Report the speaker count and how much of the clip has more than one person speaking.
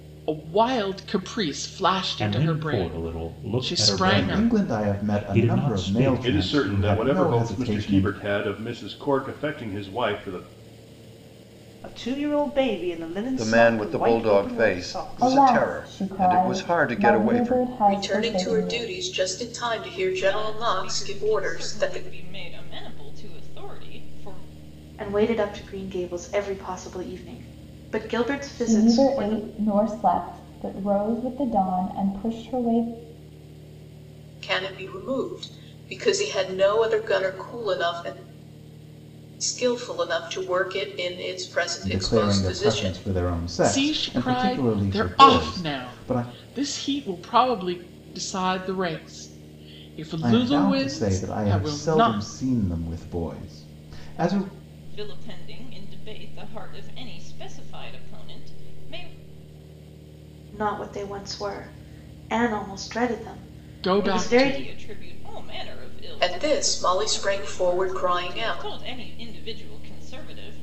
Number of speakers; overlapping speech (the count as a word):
ten, about 33%